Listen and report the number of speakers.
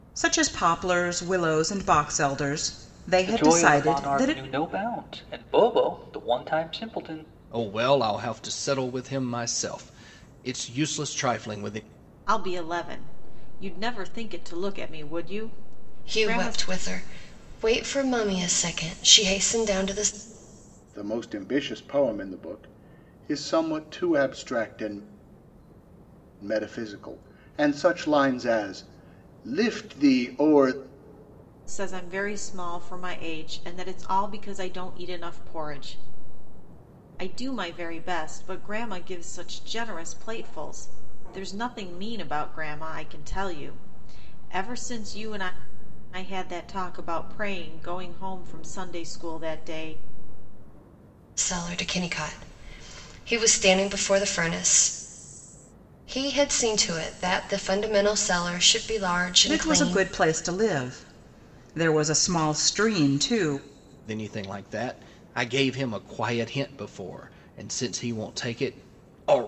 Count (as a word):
six